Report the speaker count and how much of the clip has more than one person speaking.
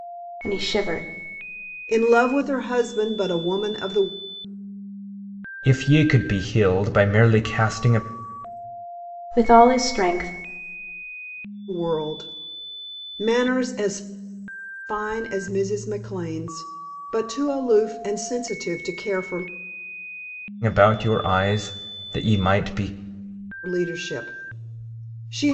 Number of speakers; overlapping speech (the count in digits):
3, no overlap